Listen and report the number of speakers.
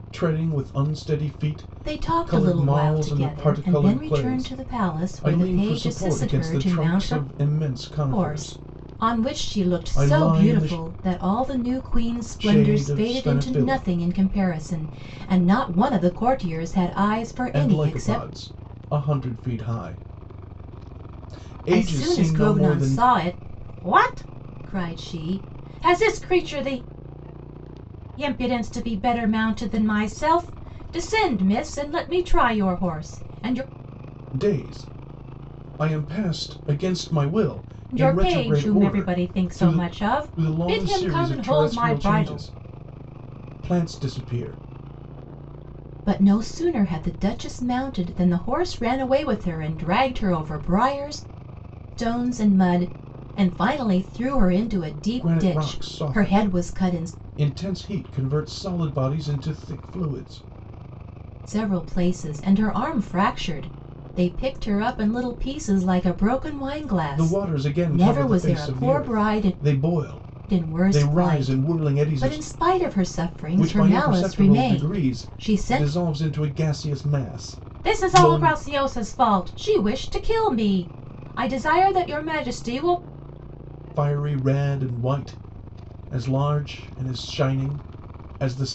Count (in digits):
2